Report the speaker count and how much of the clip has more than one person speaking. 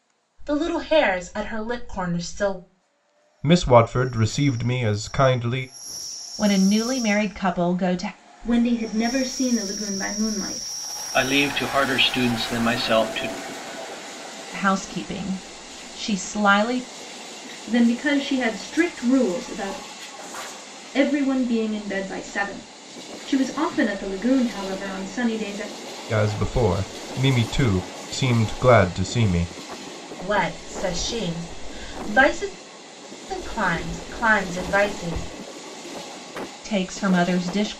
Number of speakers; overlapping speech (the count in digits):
5, no overlap